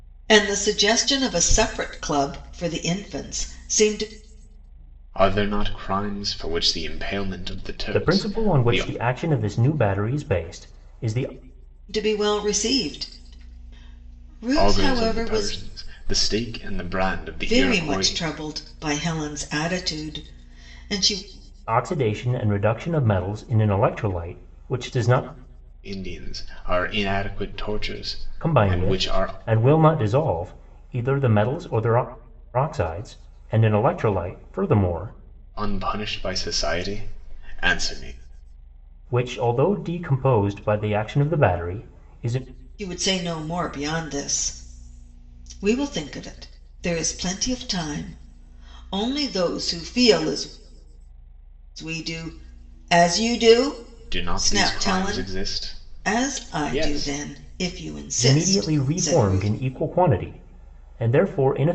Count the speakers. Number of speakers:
three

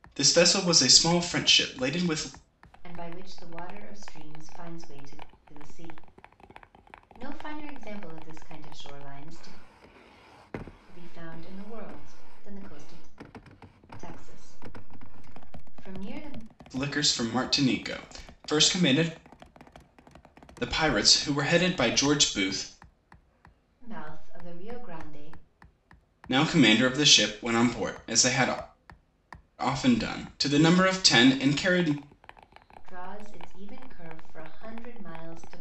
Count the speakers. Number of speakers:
two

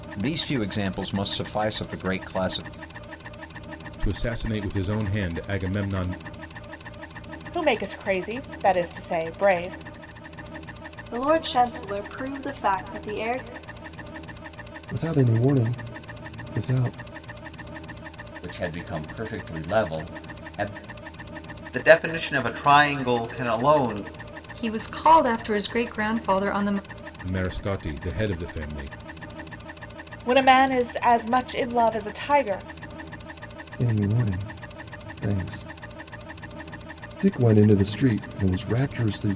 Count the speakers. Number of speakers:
eight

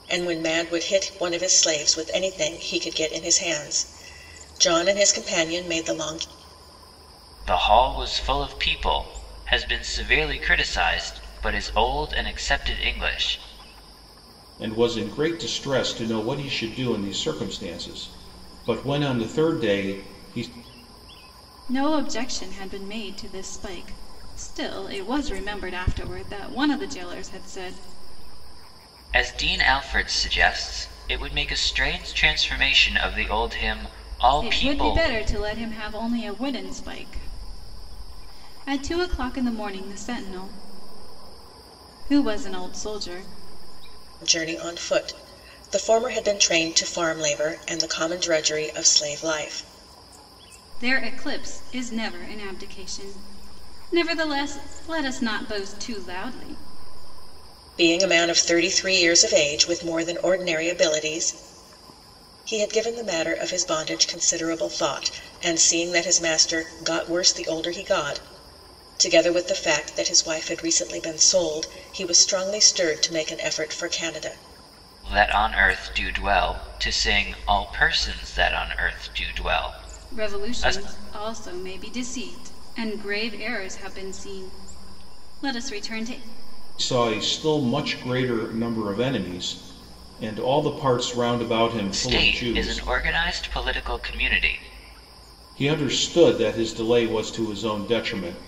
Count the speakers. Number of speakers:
four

